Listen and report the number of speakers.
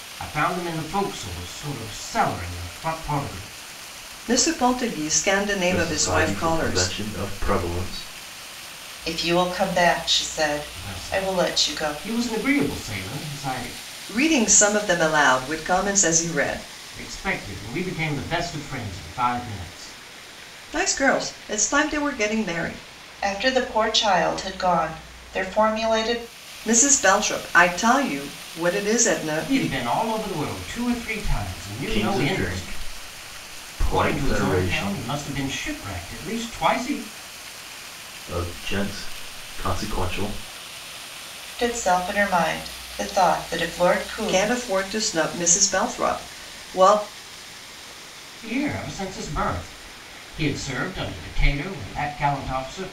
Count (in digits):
4